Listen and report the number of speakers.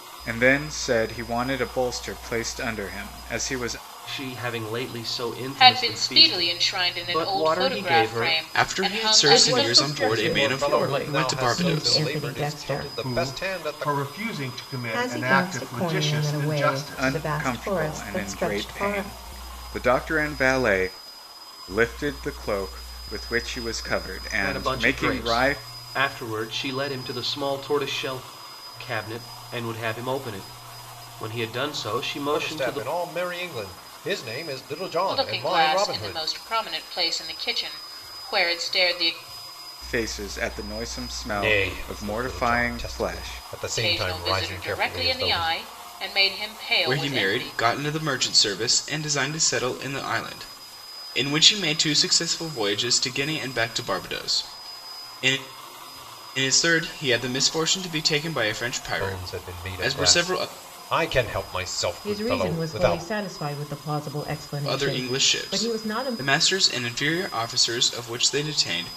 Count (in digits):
8